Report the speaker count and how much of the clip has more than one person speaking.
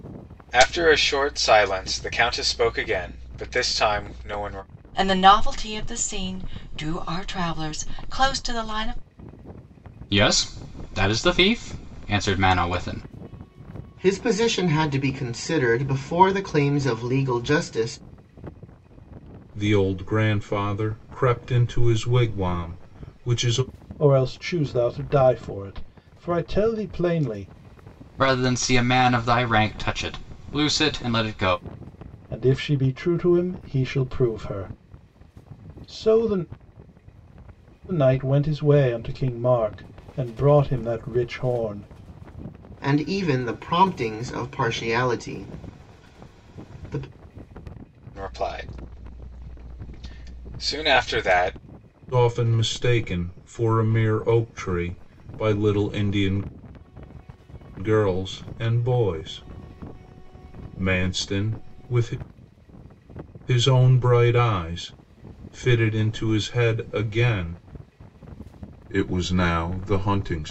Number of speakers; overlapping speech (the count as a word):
six, no overlap